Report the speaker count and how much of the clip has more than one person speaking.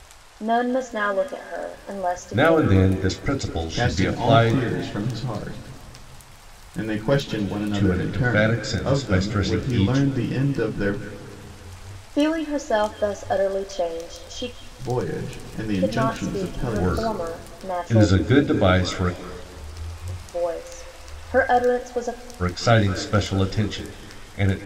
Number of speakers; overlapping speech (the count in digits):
3, about 25%